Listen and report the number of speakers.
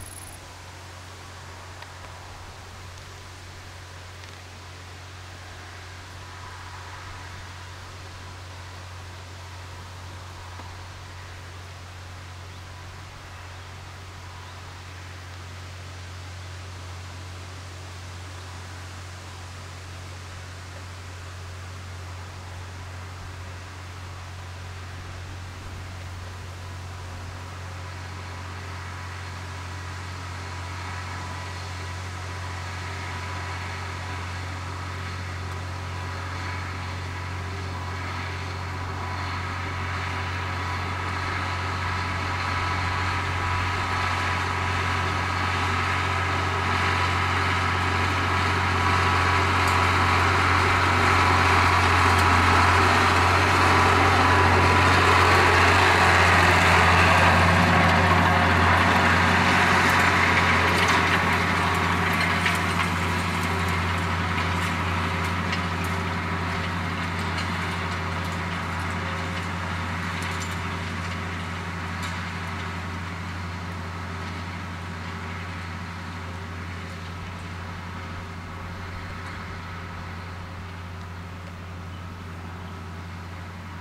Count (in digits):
0